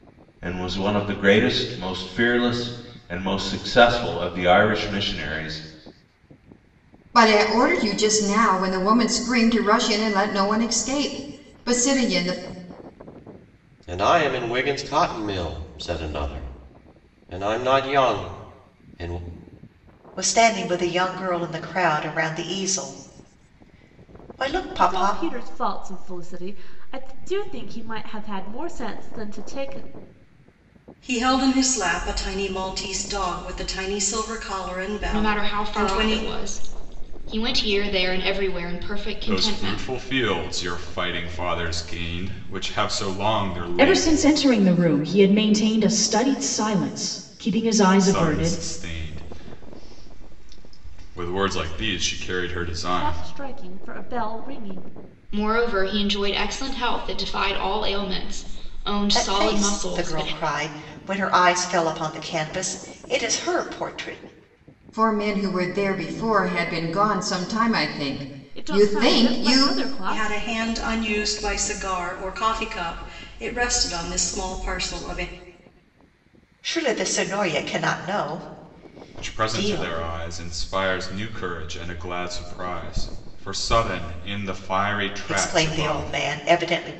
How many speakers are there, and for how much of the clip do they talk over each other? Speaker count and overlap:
9, about 10%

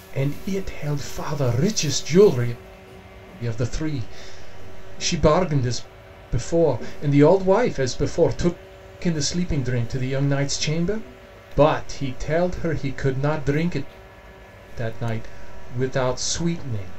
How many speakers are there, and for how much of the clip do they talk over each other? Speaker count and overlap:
1, no overlap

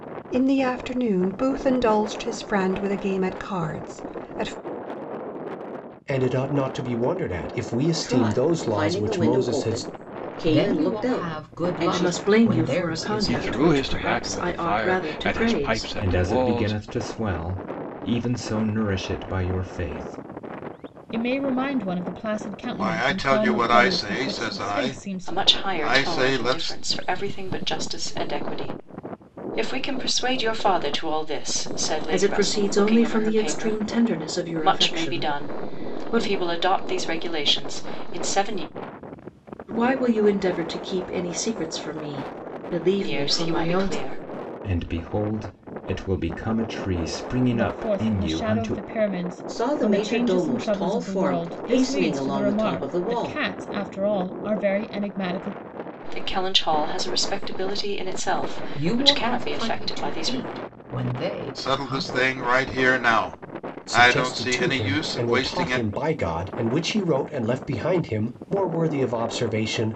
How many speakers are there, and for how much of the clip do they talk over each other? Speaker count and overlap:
10, about 38%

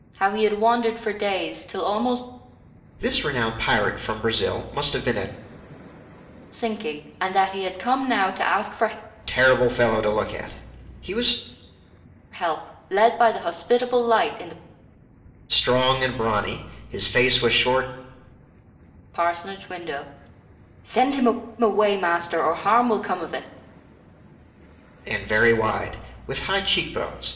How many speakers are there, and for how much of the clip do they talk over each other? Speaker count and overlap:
2, no overlap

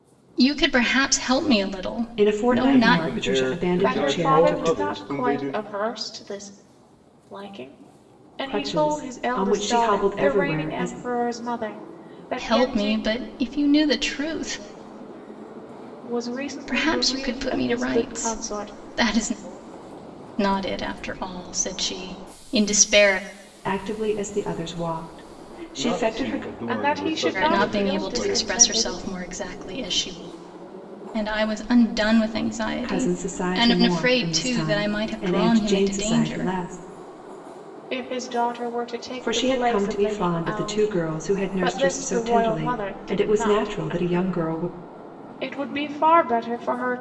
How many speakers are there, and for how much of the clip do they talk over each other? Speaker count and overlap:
4, about 45%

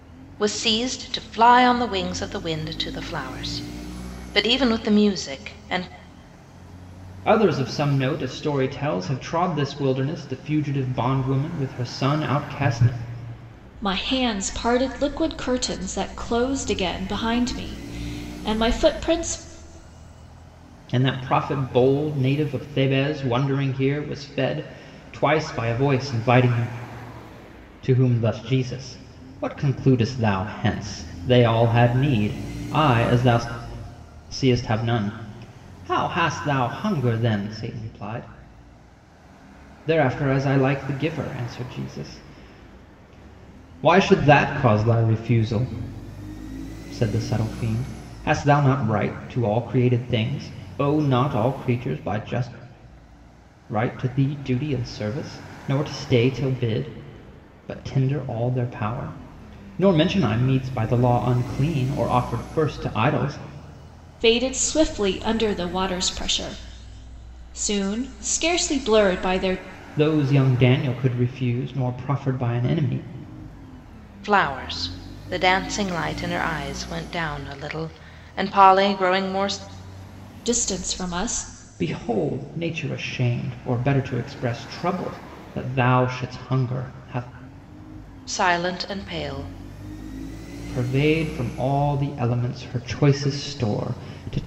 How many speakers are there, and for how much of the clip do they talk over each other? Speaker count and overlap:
3, no overlap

